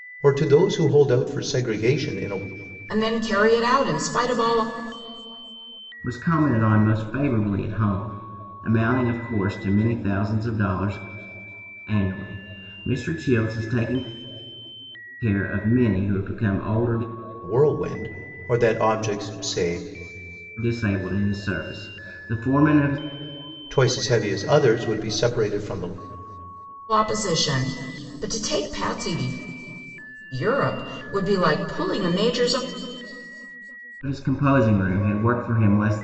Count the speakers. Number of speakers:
three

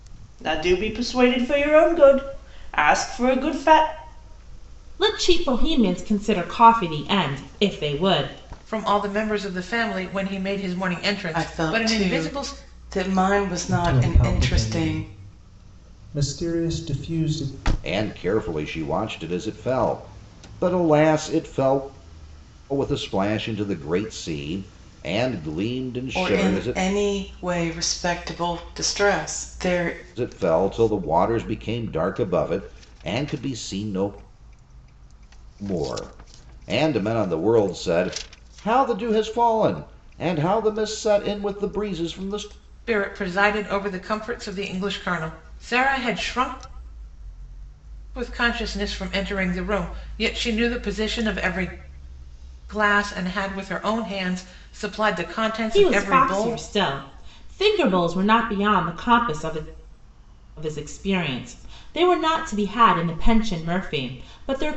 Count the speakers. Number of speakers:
six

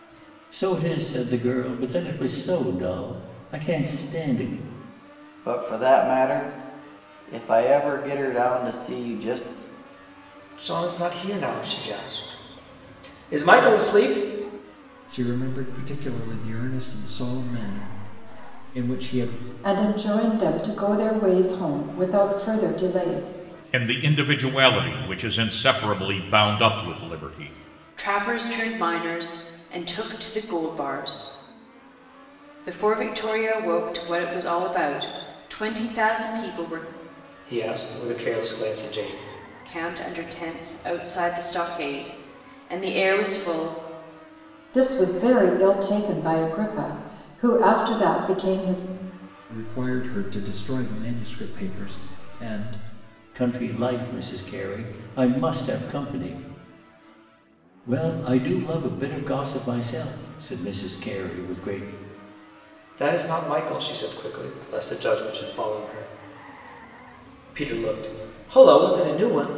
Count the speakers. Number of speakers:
seven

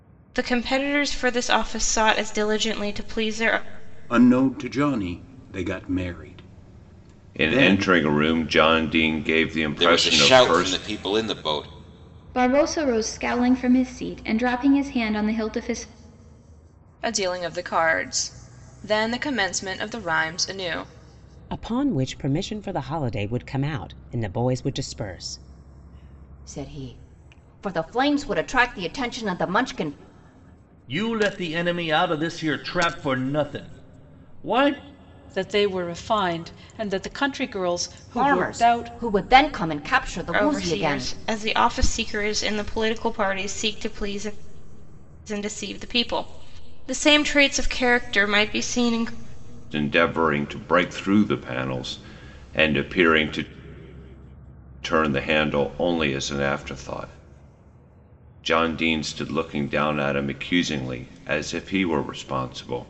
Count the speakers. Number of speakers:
ten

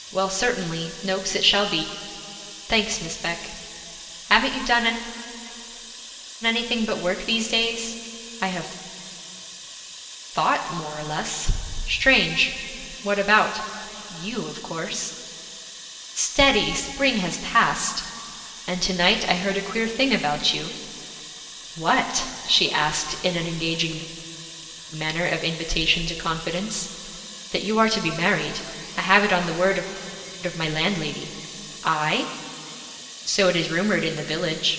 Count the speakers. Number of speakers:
one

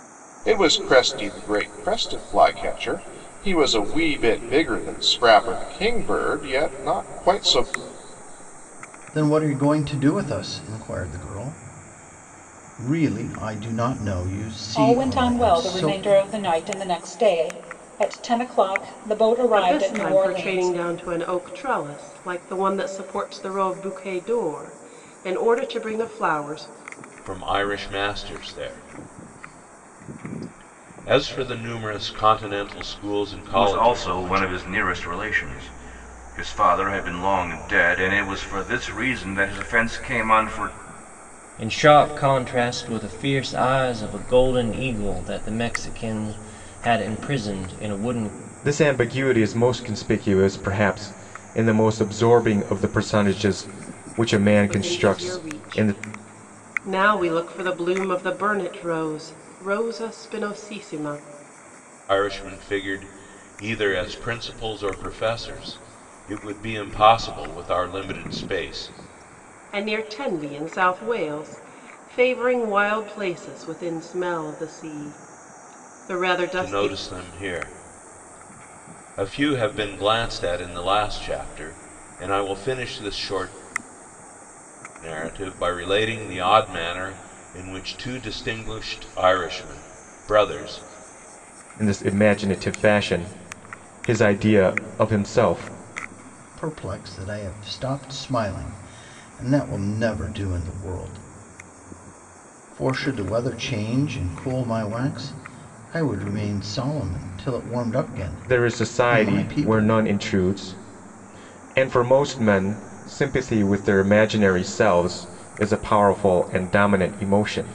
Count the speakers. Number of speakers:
eight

